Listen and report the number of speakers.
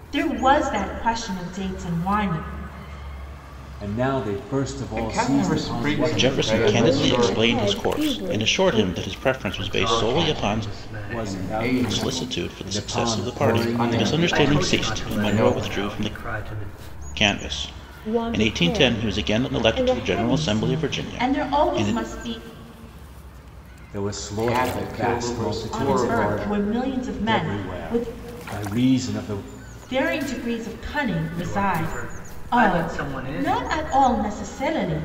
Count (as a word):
six